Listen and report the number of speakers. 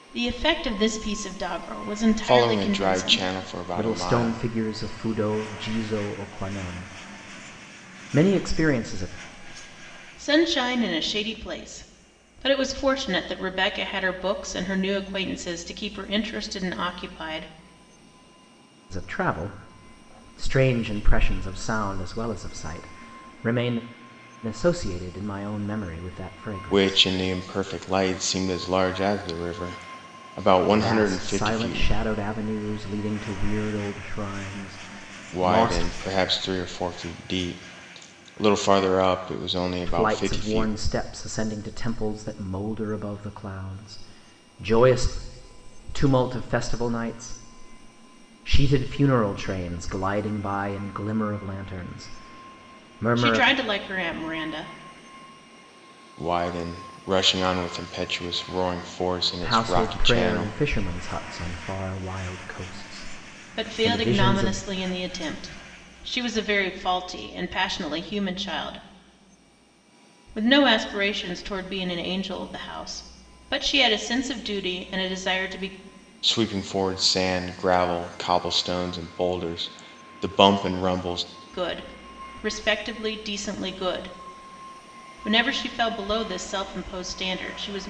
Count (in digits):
3